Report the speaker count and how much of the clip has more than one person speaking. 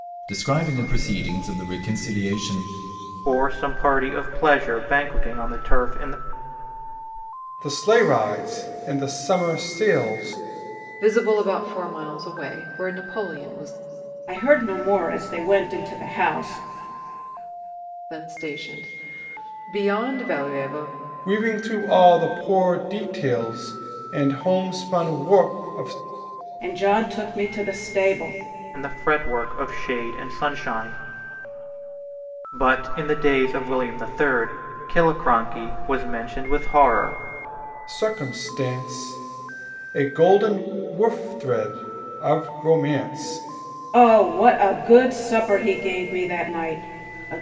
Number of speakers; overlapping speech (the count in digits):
5, no overlap